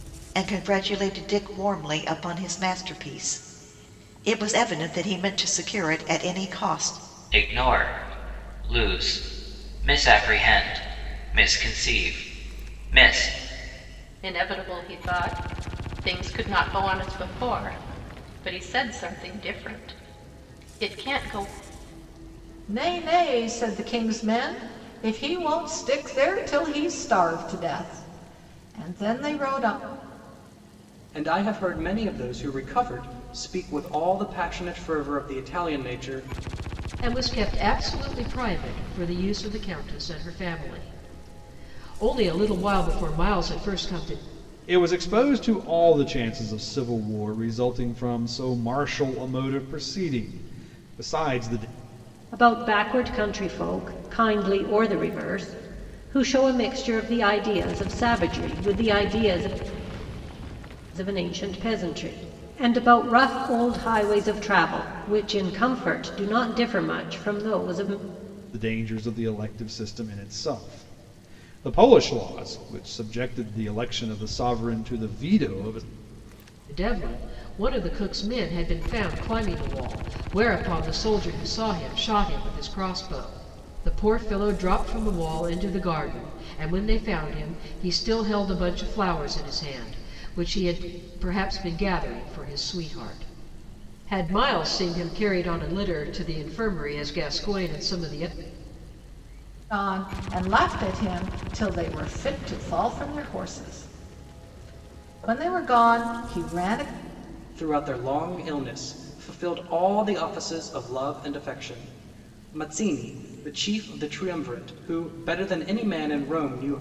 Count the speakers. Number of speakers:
8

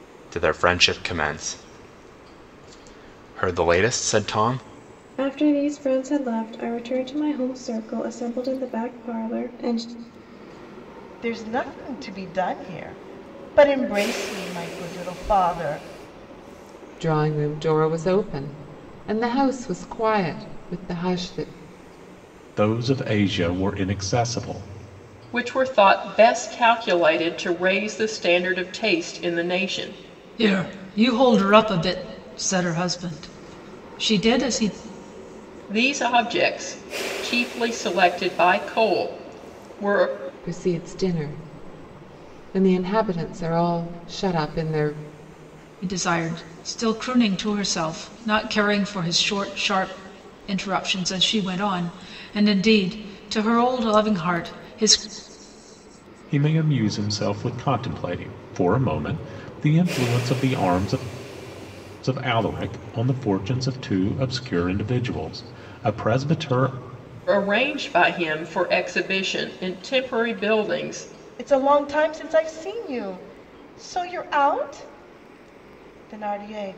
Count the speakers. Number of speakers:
7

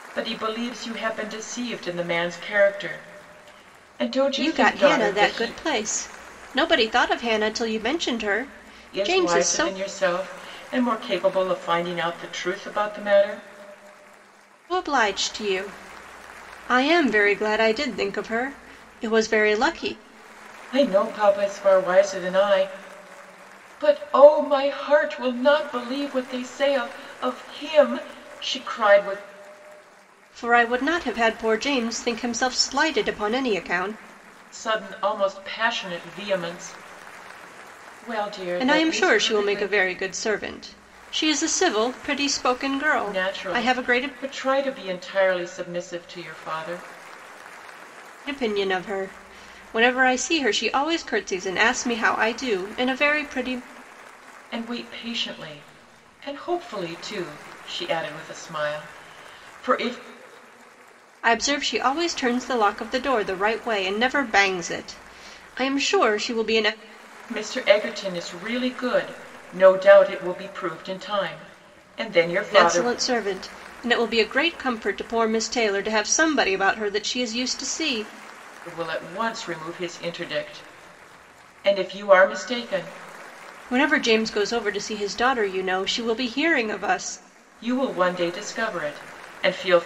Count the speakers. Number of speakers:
2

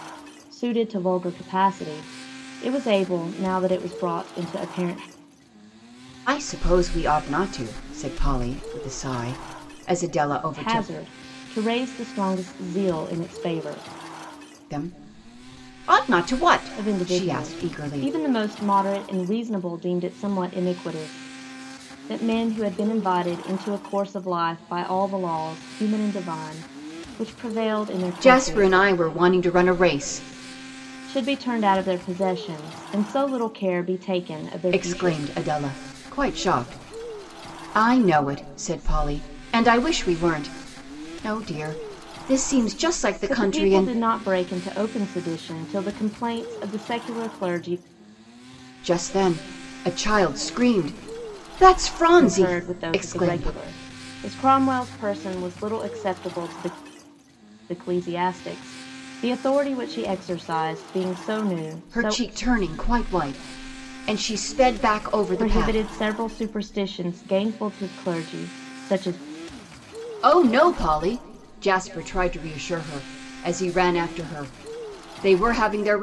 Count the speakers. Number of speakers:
2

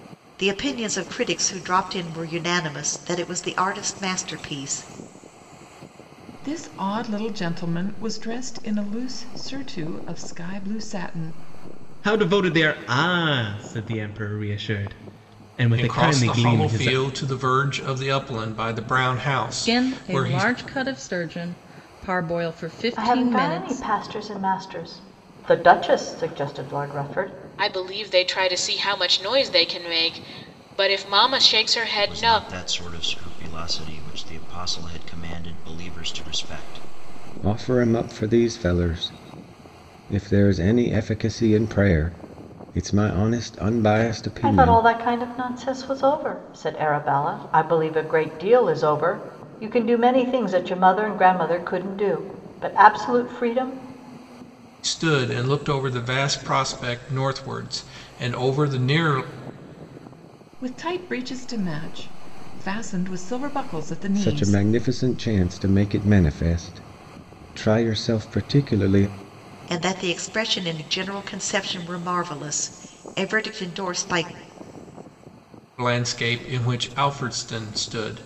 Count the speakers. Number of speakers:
9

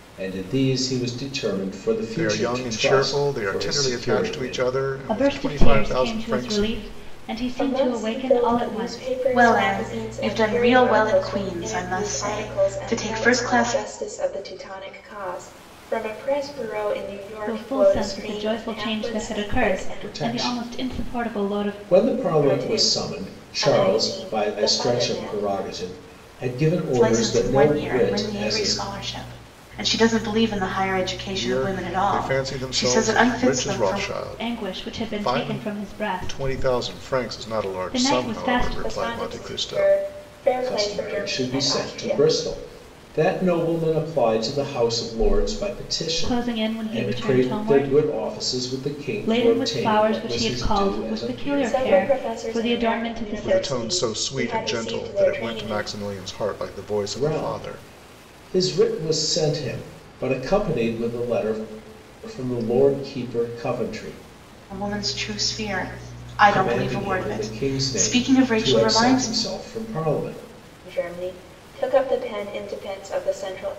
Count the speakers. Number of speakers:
5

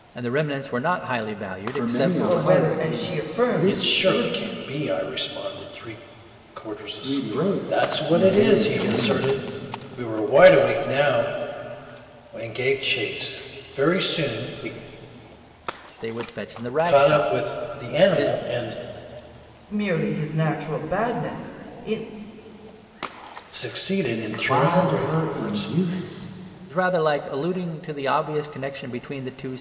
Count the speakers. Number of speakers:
4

